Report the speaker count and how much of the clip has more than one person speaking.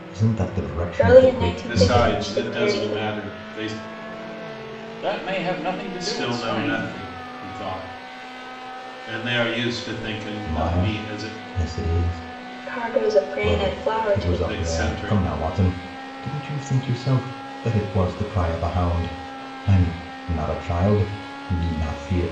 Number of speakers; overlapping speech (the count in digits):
4, about 26%